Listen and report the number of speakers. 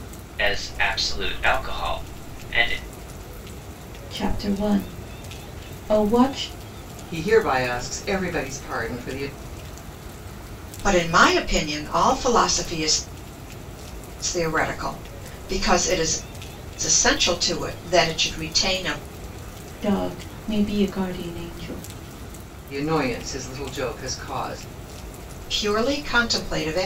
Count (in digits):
4